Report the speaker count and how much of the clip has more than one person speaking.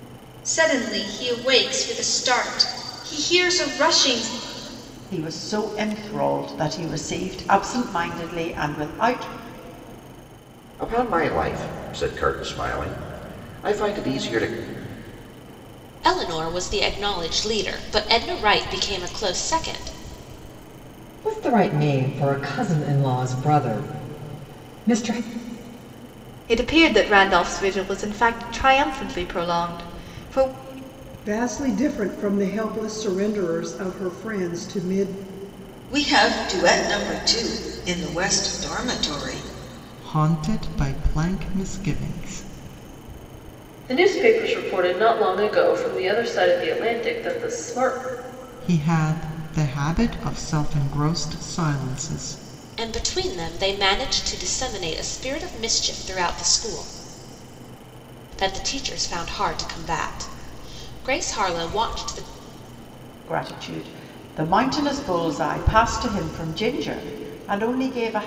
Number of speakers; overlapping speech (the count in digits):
10, no overlap